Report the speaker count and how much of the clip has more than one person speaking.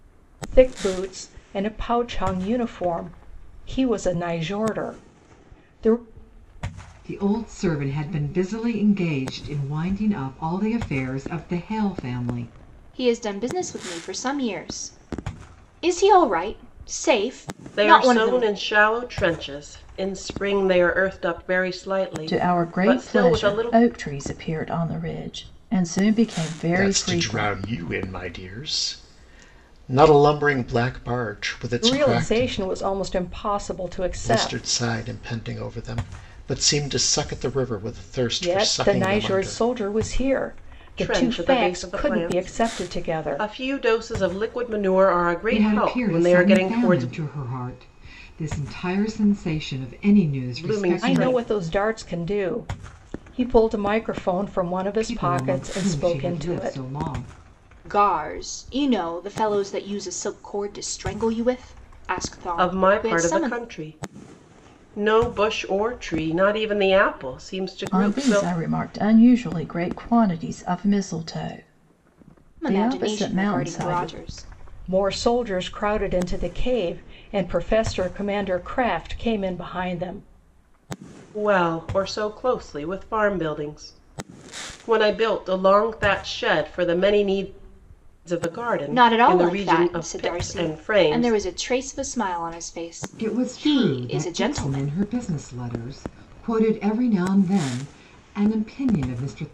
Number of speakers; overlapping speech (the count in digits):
6, about 21%